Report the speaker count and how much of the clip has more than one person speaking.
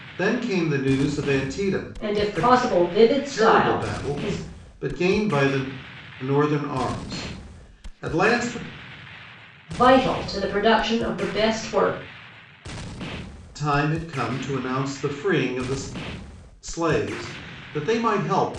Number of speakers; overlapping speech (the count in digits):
2, about 9%